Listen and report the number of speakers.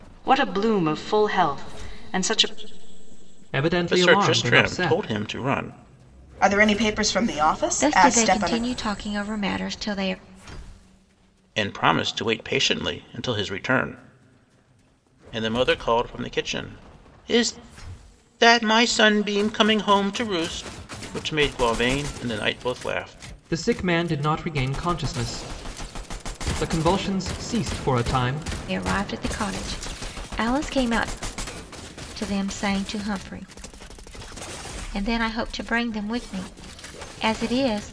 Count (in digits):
5